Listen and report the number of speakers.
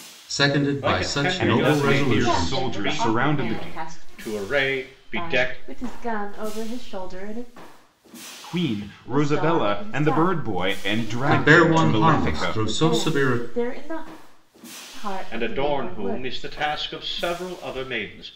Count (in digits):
4